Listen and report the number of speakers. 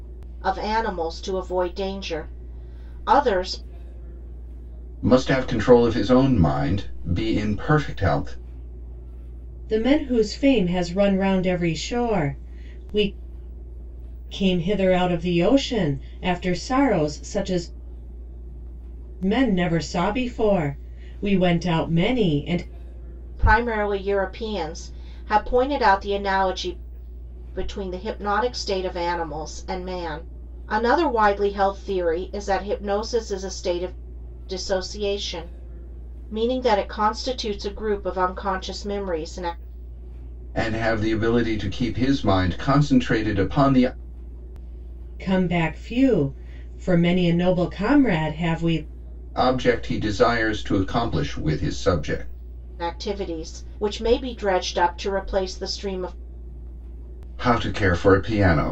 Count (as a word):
three